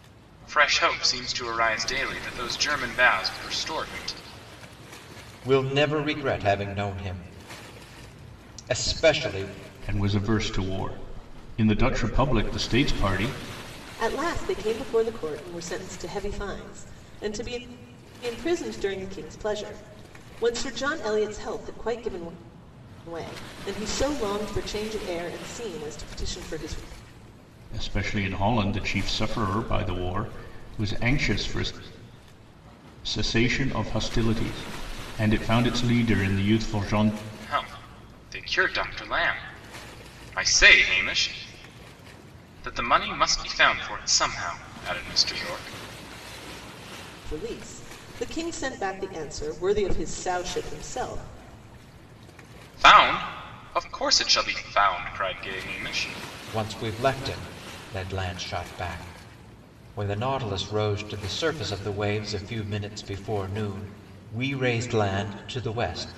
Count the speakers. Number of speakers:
4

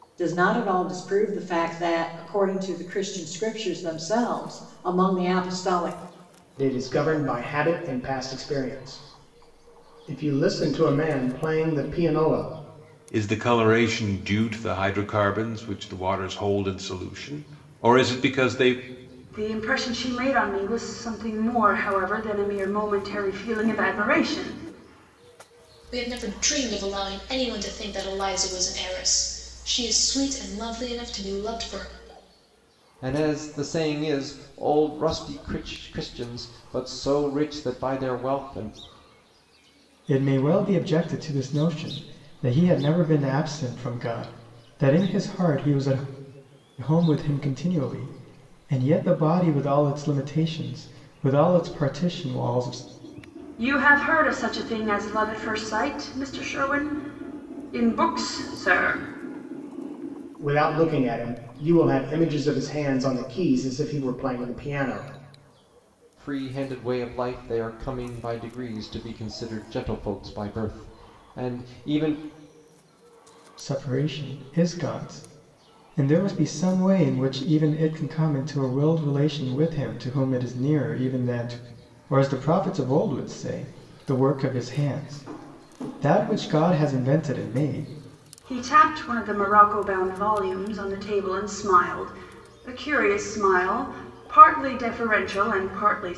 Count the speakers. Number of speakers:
7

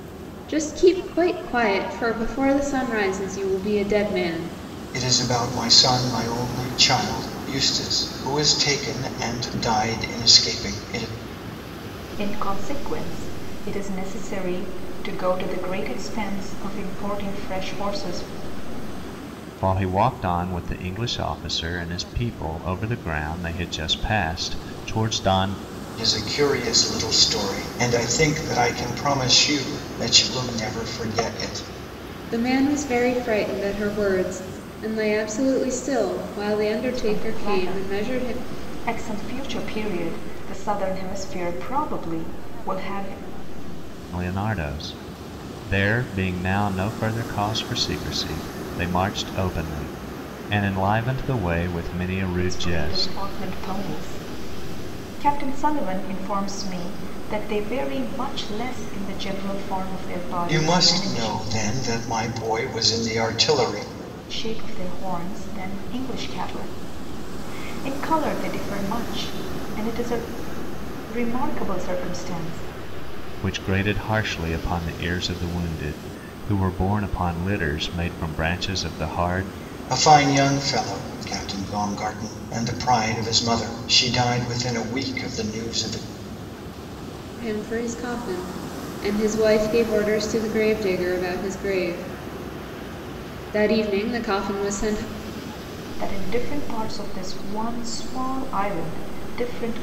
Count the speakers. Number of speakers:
4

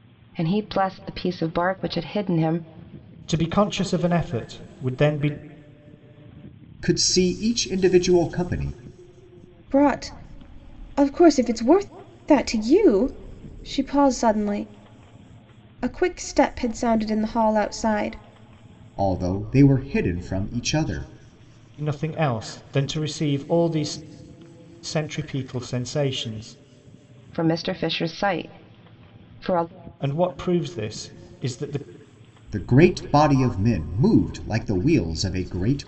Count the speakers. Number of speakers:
4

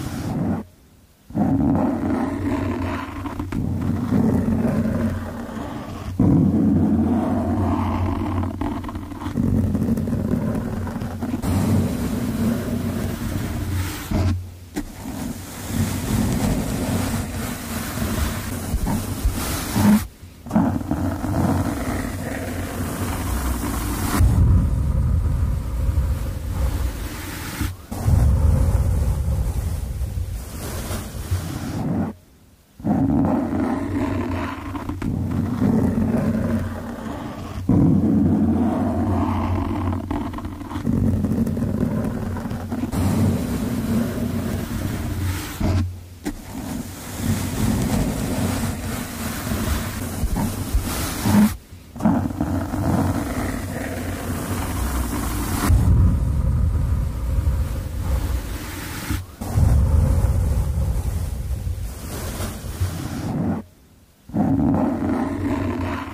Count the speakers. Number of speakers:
0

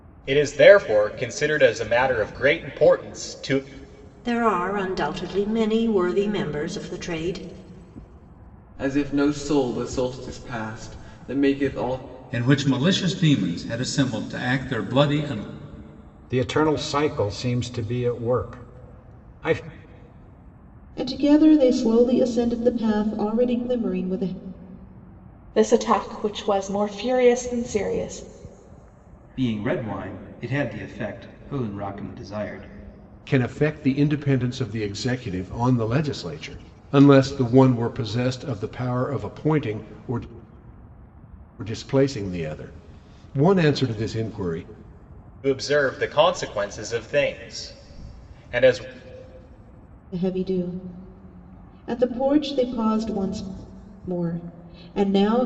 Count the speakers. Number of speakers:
9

